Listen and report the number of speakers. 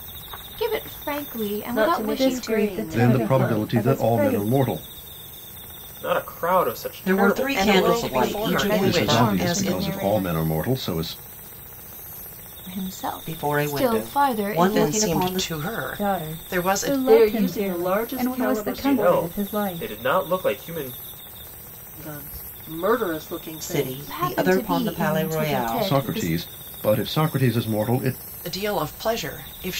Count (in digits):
7